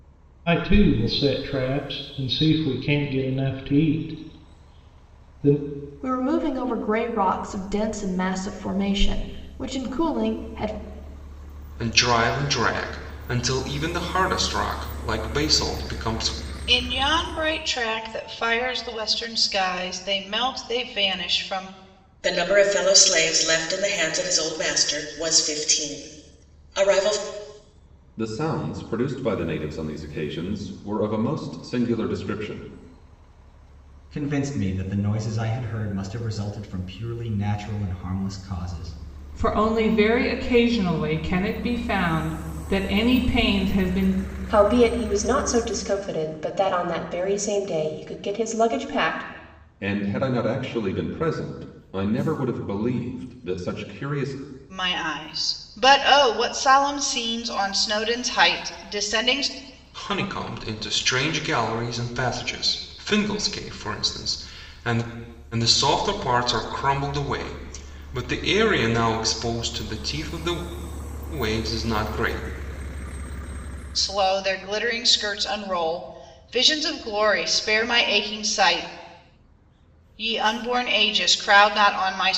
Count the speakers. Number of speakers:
nine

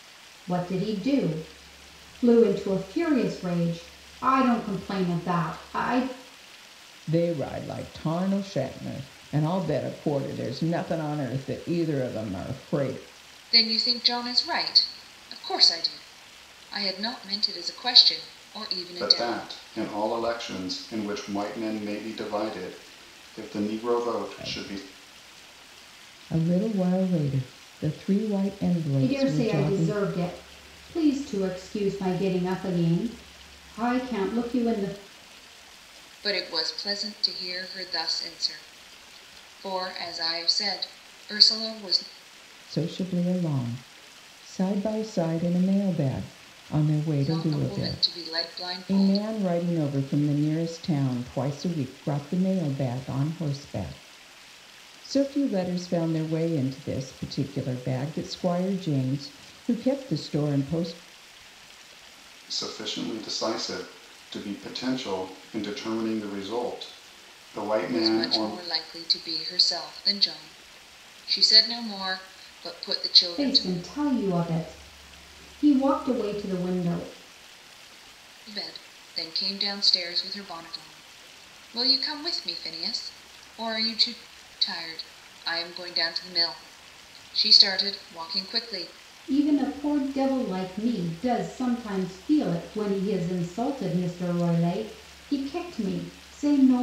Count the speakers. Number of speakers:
four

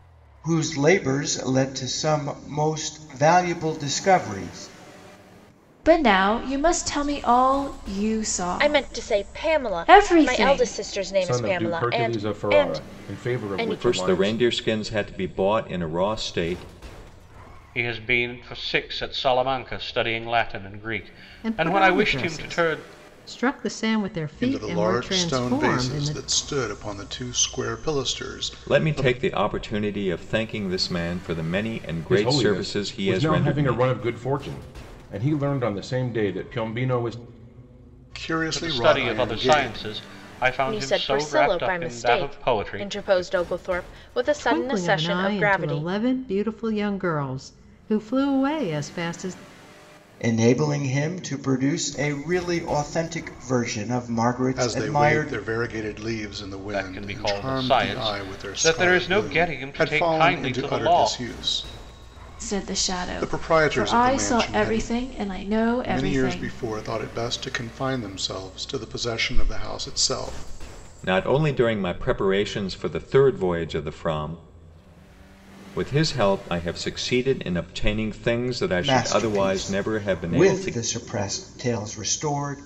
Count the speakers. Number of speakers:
eight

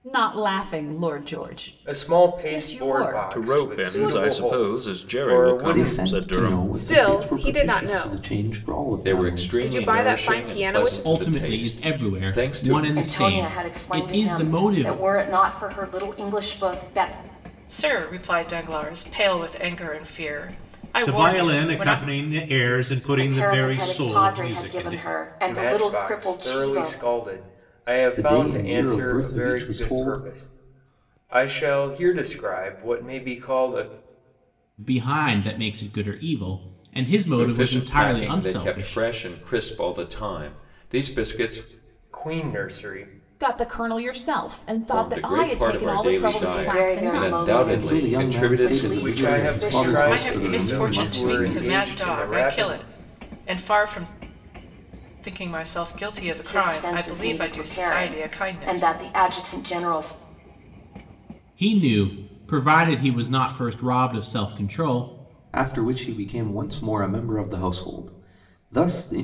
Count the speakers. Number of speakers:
ten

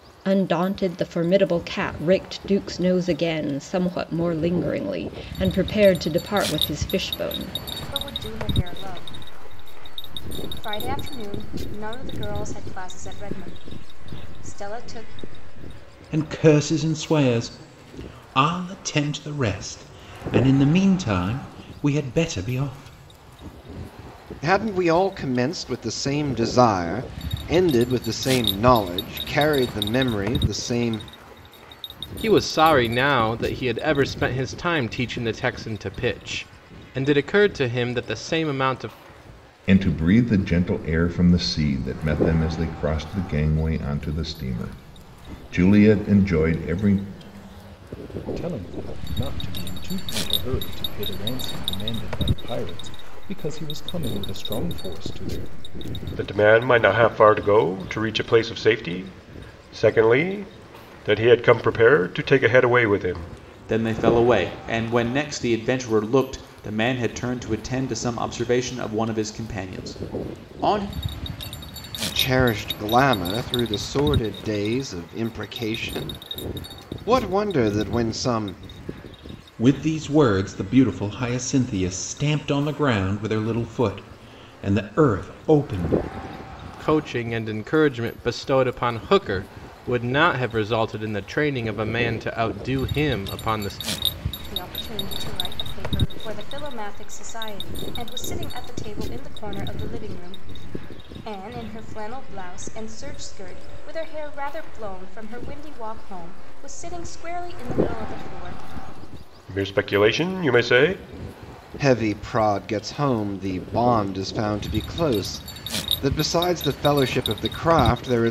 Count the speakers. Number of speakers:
nine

